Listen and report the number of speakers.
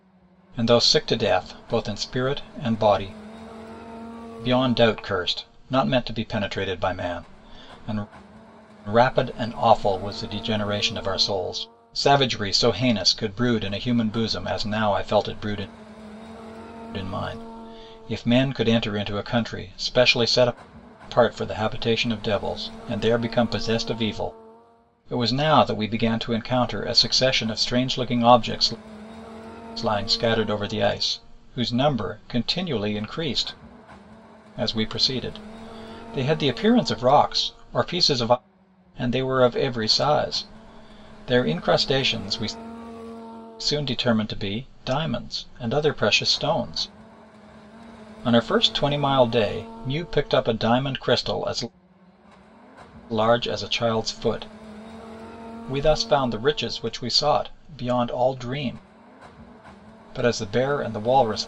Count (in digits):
1